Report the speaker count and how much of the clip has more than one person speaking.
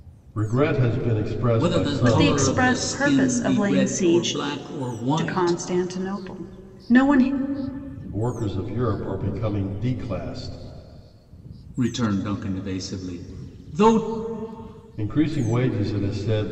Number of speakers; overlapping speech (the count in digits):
3, about 20%